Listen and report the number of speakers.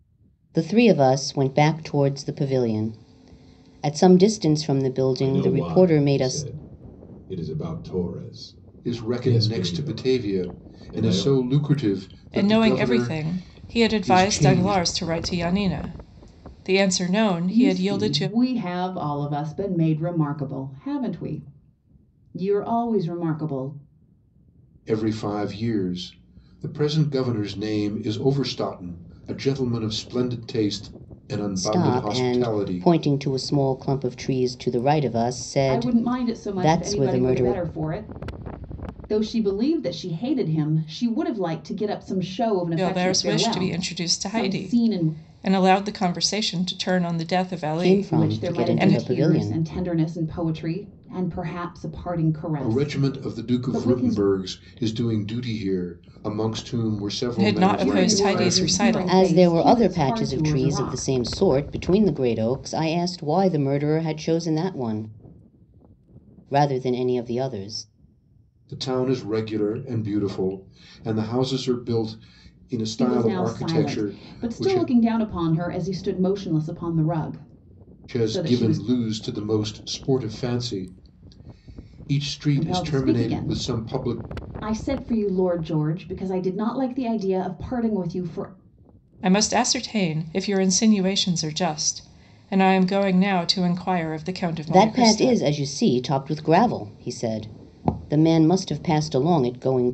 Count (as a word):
five